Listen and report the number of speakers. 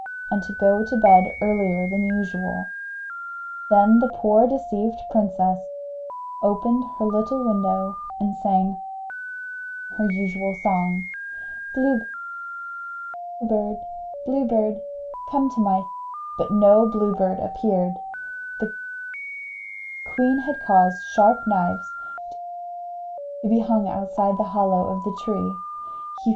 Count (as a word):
one